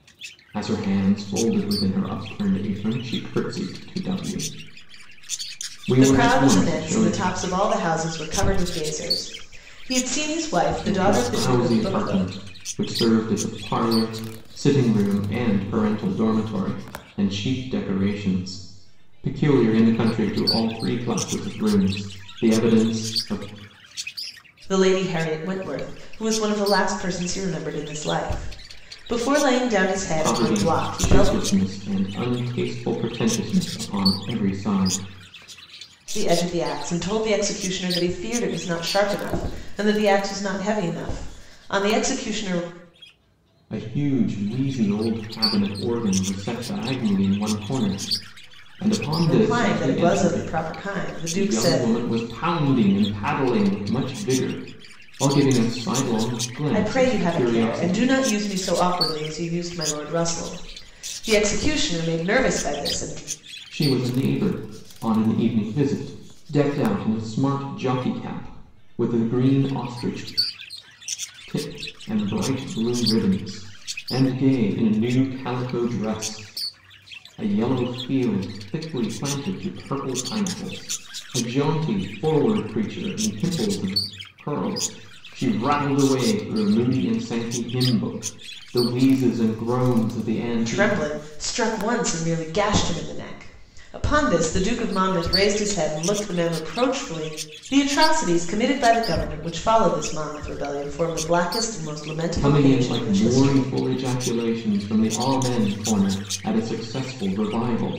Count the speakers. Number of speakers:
2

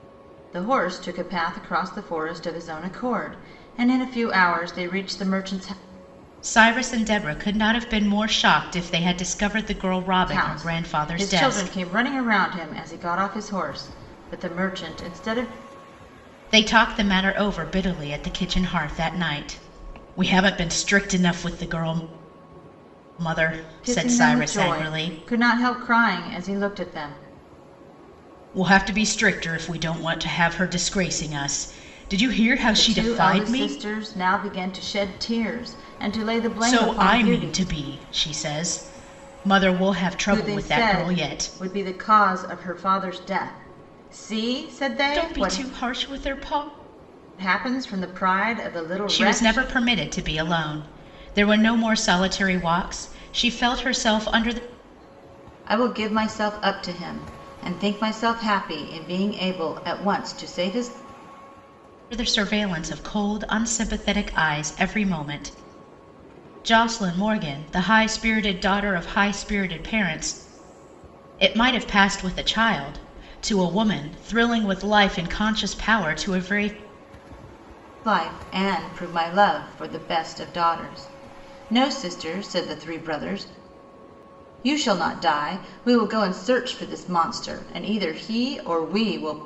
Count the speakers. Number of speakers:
2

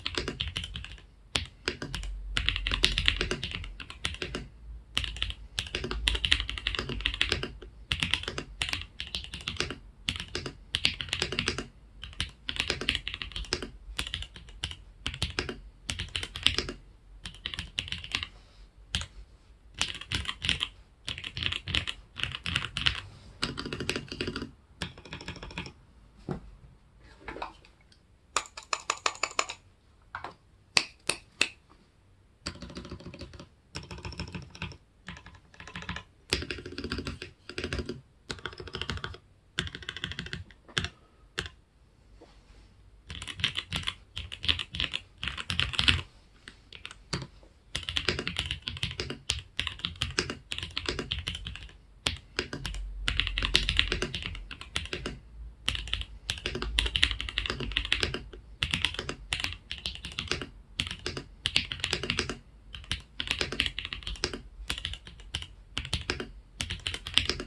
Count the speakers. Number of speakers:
0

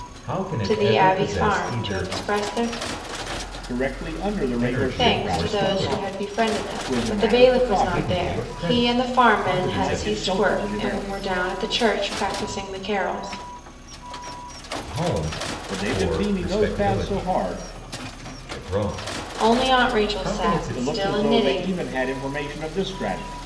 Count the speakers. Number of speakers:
3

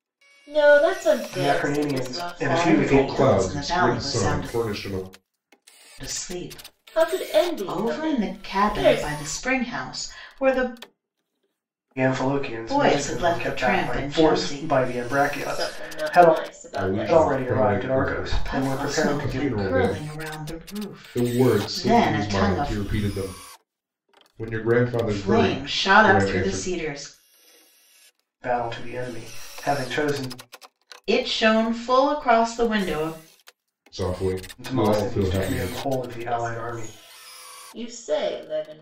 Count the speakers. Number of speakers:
4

